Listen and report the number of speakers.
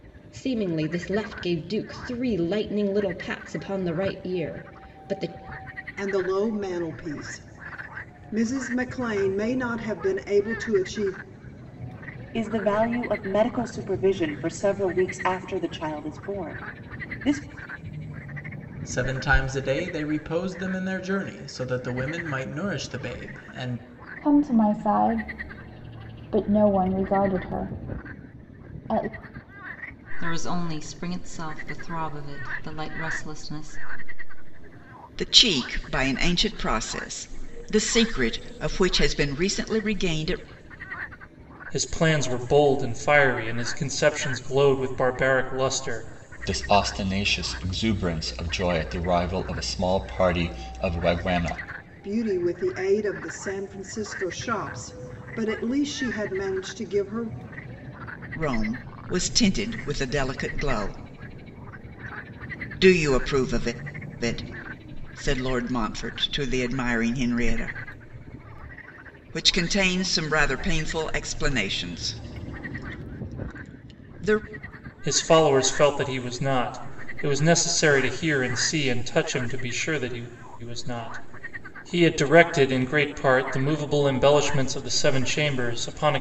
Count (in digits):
9